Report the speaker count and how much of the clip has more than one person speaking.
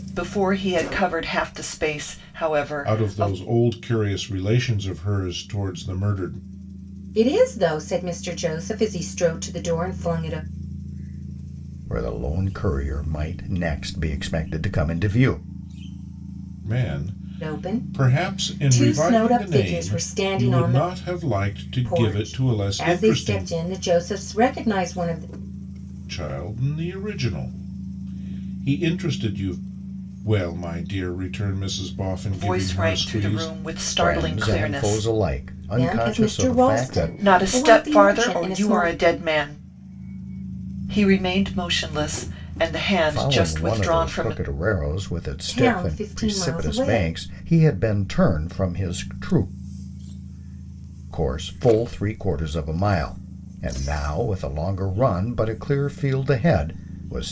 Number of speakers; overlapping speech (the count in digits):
4, about 25%